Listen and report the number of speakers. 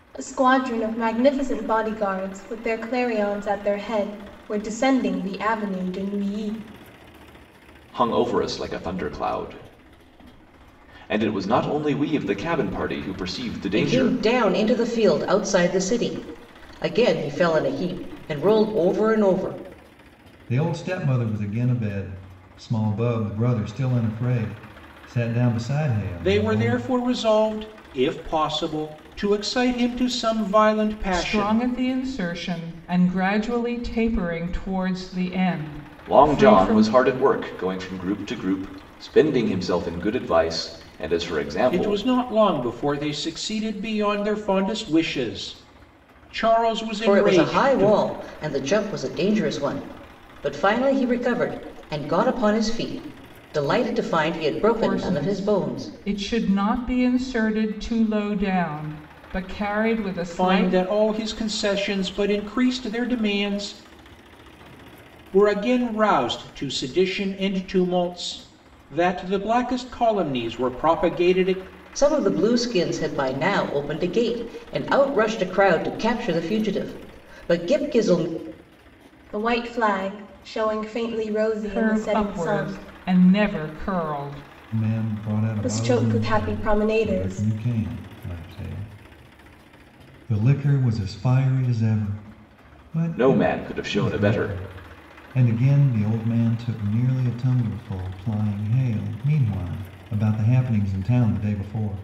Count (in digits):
6